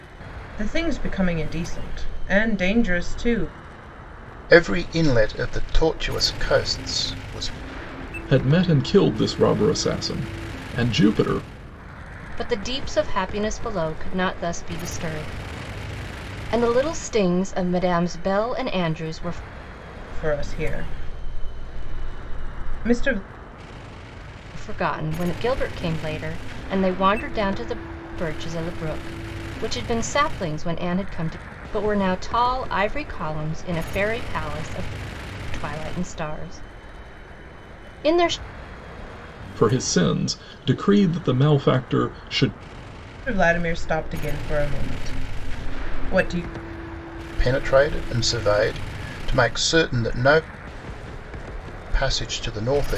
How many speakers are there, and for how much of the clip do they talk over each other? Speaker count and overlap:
four, no overlap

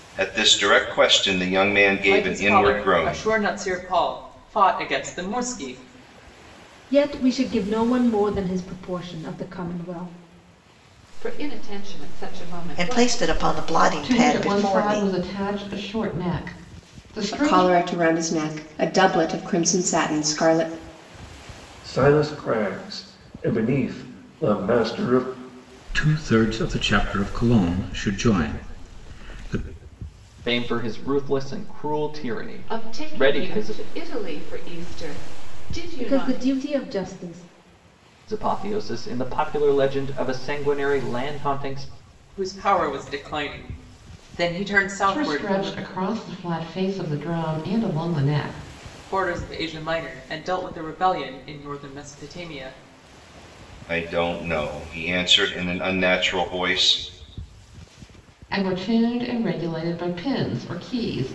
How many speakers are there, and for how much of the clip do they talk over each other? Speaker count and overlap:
ten, about 10%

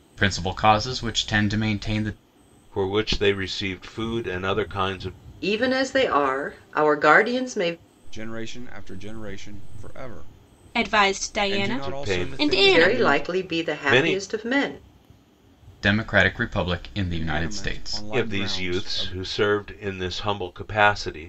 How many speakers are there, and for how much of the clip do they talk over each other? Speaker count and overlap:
five, about 22%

